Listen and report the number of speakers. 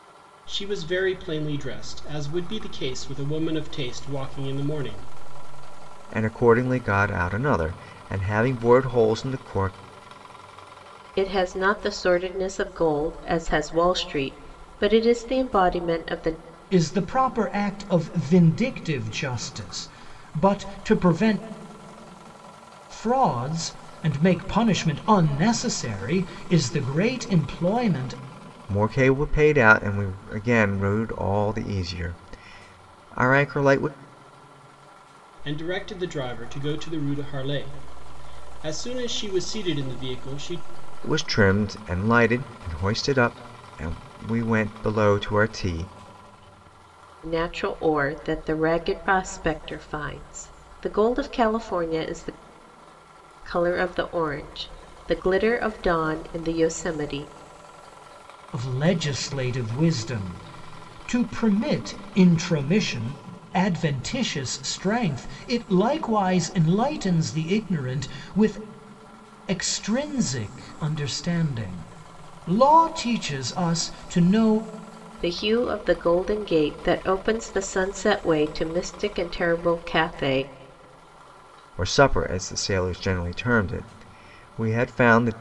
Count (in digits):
4